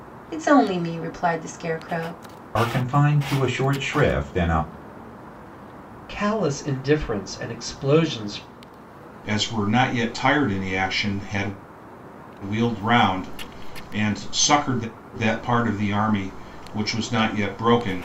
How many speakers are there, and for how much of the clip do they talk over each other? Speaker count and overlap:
4, no overlap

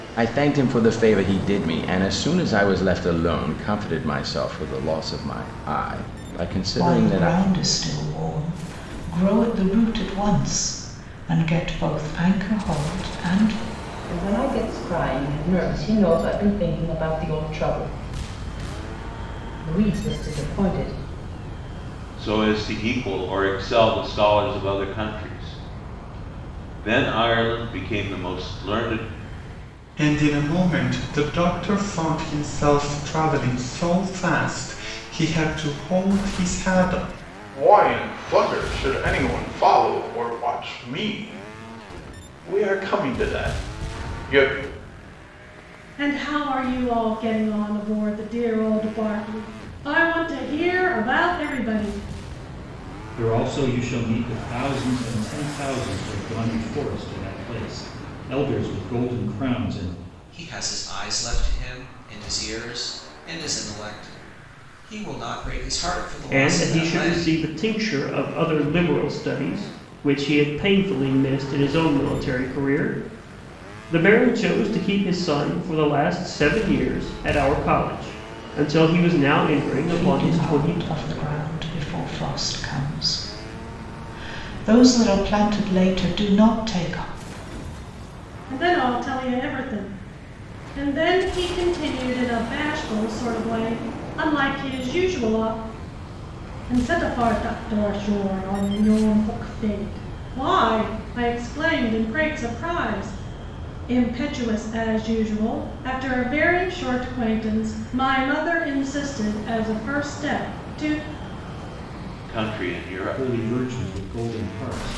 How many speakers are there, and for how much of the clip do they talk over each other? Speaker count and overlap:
10, about 3%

